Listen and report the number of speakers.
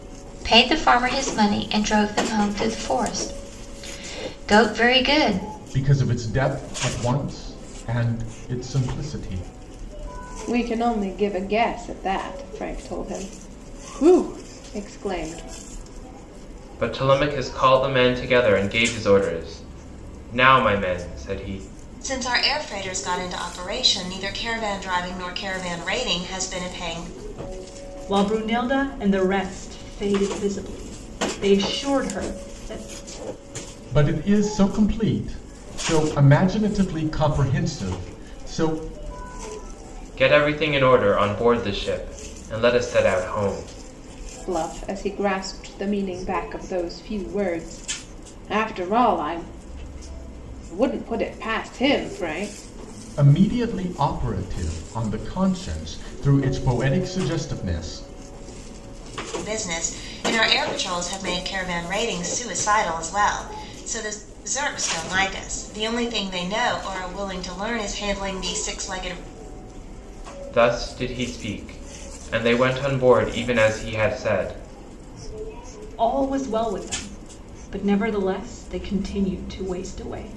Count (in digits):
6